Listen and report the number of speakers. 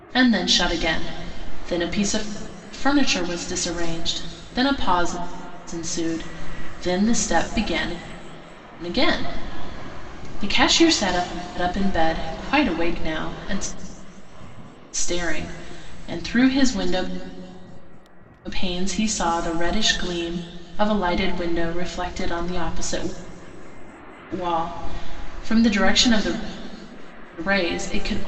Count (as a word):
one